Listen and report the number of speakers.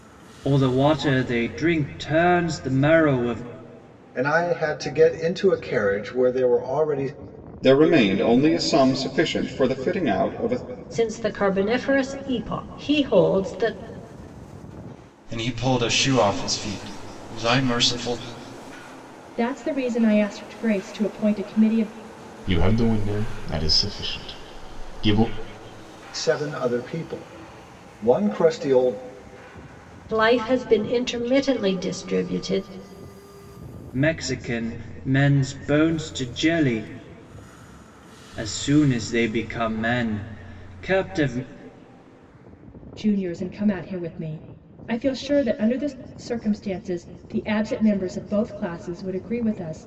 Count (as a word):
seven